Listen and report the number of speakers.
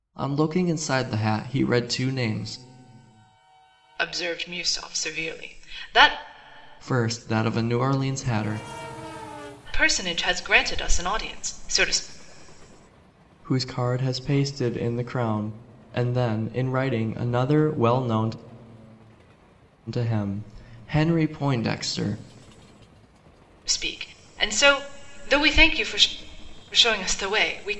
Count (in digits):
2